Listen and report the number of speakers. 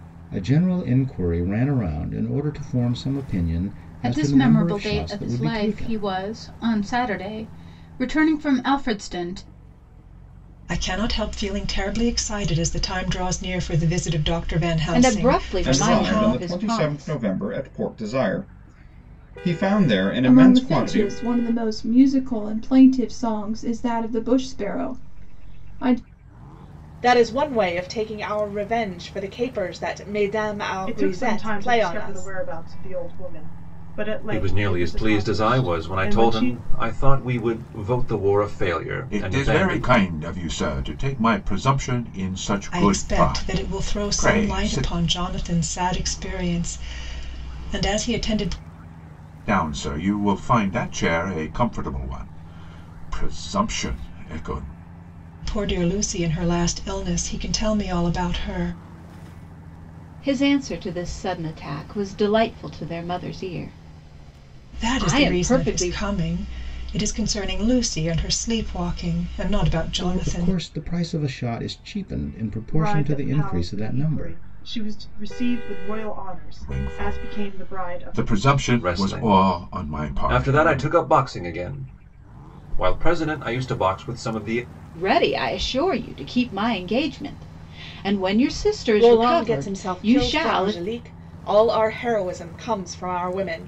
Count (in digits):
10